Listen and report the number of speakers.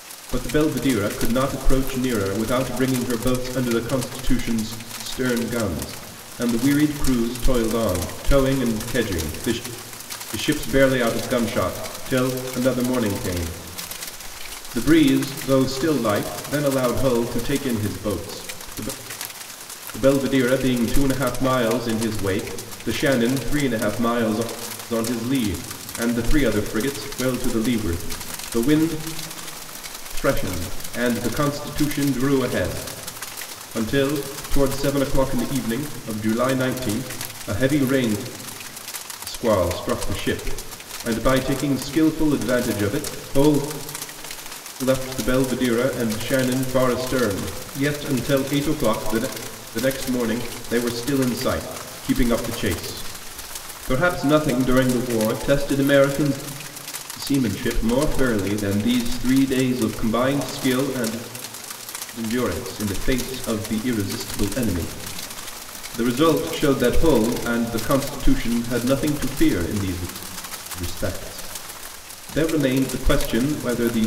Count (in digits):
1